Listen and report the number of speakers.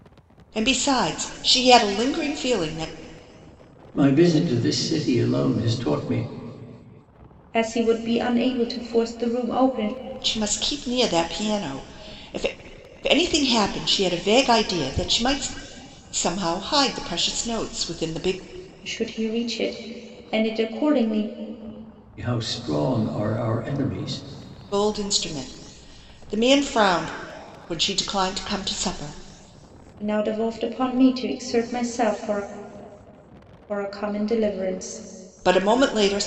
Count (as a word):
three